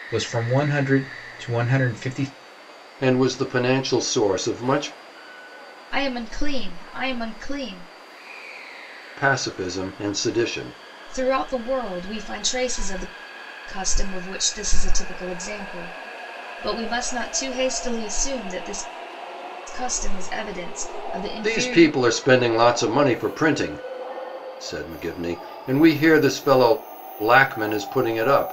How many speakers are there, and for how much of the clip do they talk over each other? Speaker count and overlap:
3, about 2%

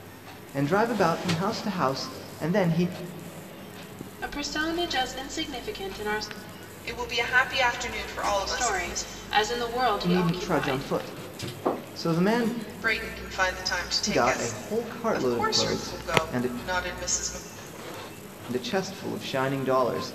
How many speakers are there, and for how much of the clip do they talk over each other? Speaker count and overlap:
3, about 17%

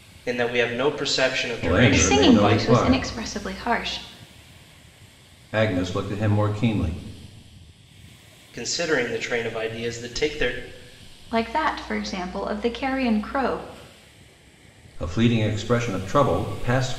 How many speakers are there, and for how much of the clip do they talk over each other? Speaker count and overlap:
3, about 9%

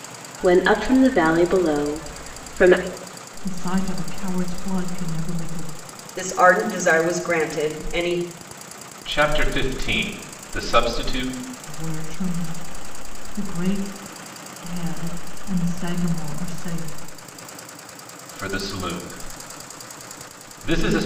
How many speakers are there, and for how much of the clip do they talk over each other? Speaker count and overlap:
4, no overlap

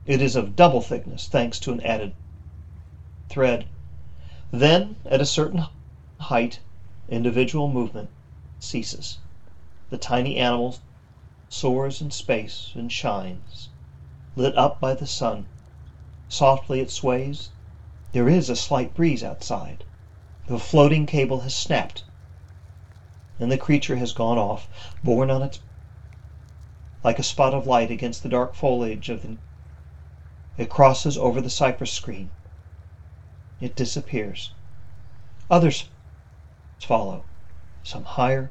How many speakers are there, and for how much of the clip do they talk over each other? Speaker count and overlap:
1, no overlap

